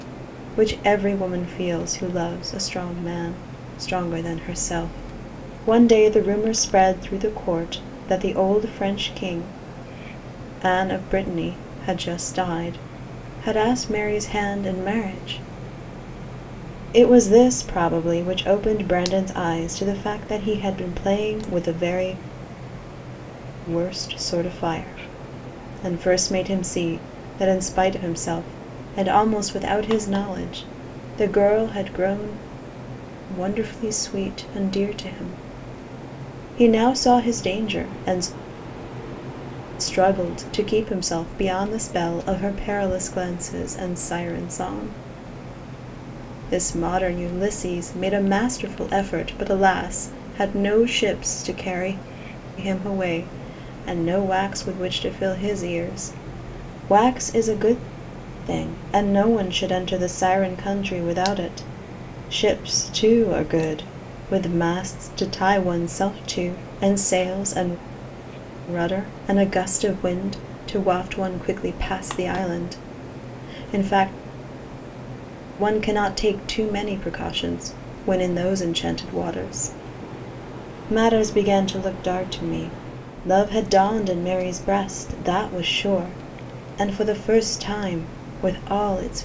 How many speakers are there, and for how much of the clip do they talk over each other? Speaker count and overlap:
1, no overlap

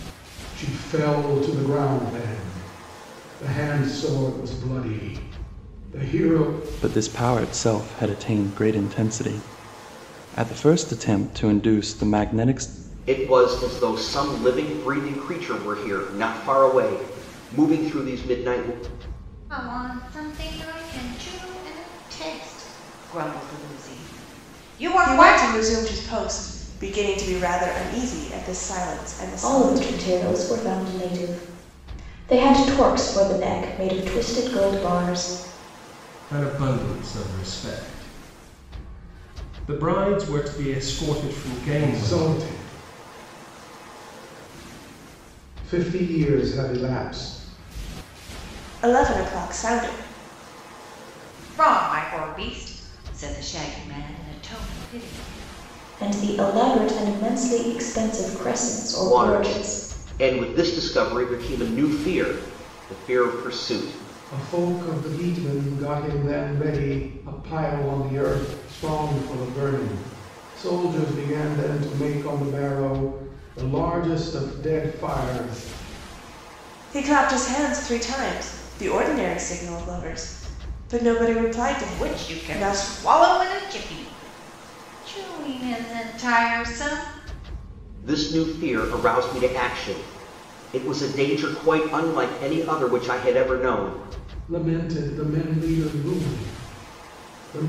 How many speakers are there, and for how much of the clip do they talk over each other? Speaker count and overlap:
7, about 4%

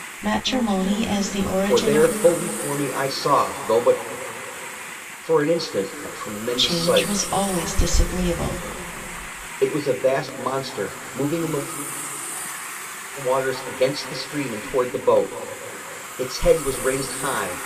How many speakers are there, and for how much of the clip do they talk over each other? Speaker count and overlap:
2, about 7%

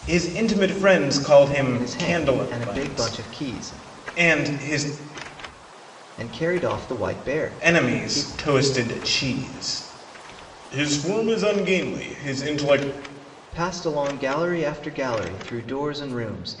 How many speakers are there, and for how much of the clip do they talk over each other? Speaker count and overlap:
2, about 16%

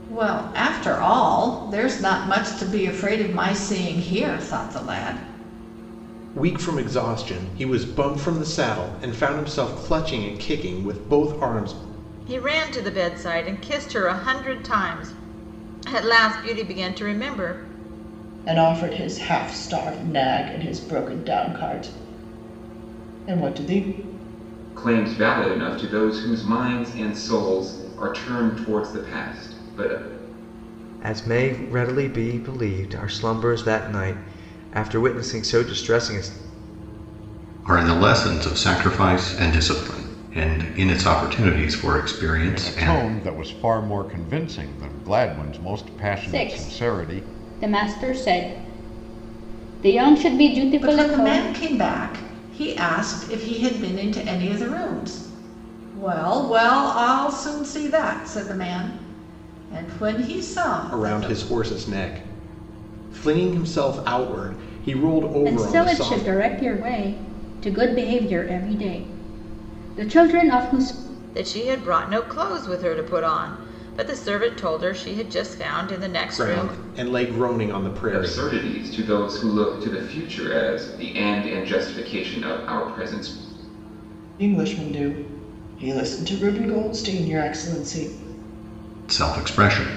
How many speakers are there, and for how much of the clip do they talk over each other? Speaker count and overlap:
9, about 5%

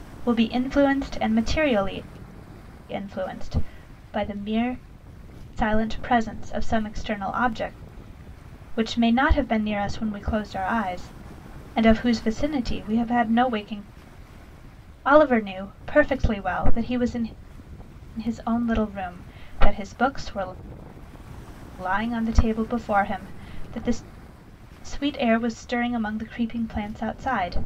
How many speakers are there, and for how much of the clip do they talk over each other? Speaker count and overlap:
1, no overlap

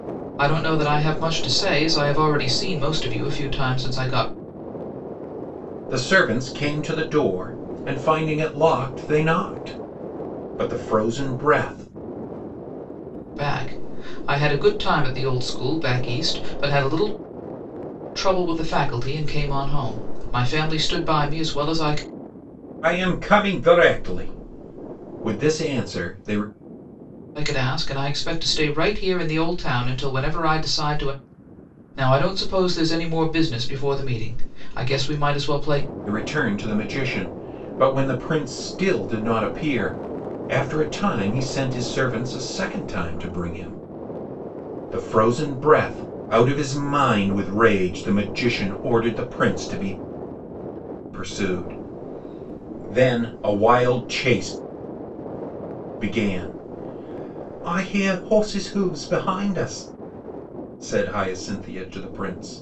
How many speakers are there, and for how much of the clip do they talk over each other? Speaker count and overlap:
2, no overlap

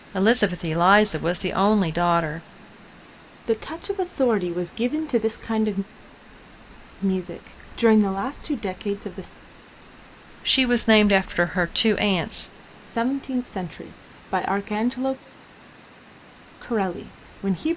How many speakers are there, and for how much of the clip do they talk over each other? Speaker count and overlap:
2, no overlap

